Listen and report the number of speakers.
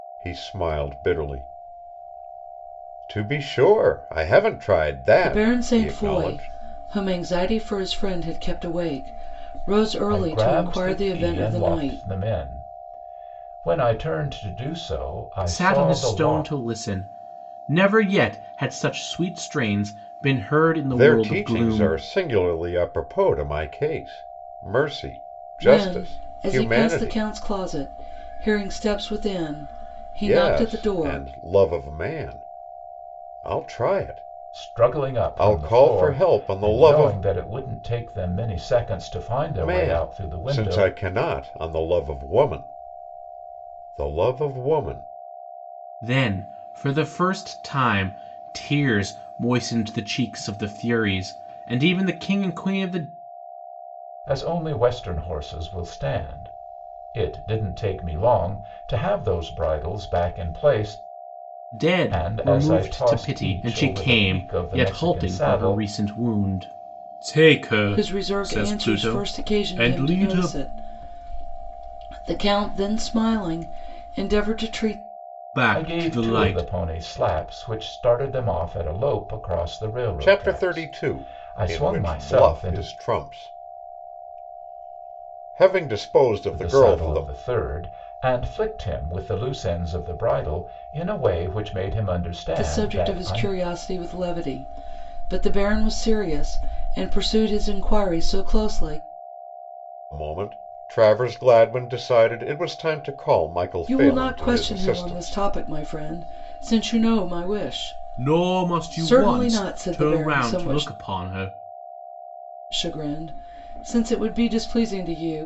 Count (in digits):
4